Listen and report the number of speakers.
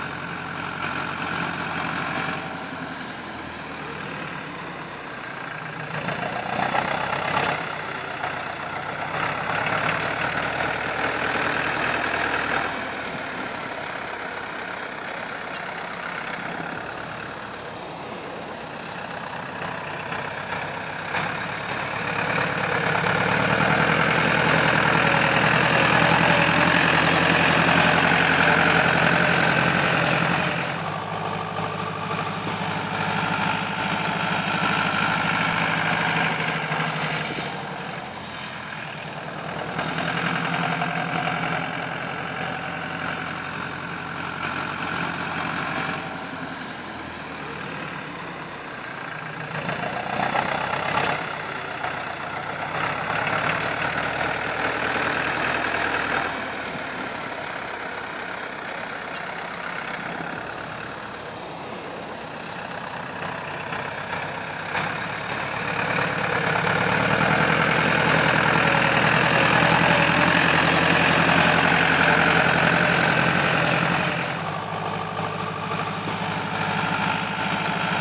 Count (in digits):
0